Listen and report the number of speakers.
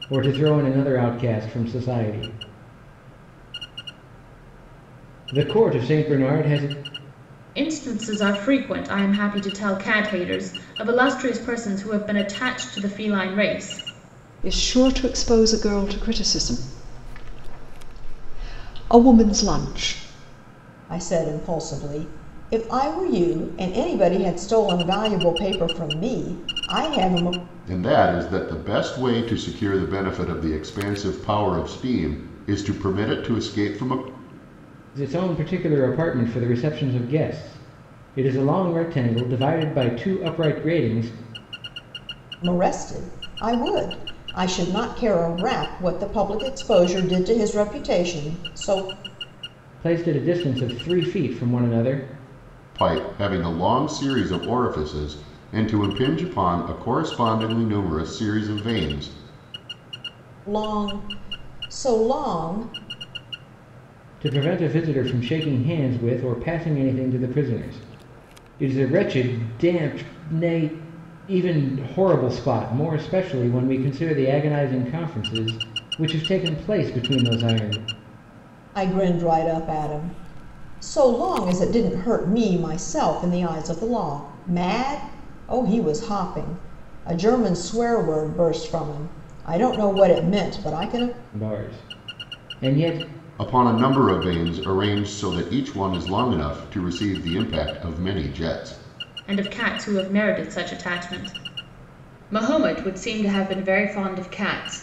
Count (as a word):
five